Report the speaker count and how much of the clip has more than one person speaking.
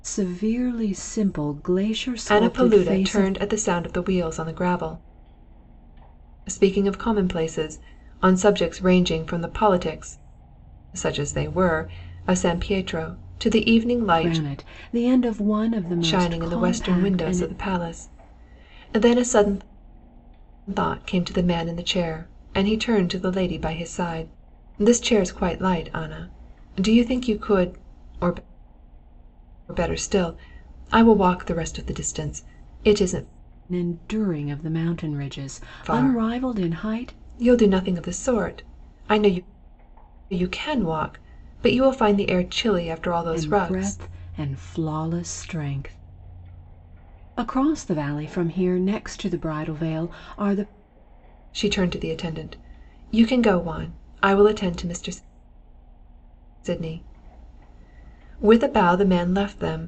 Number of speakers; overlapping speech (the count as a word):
two, about 8%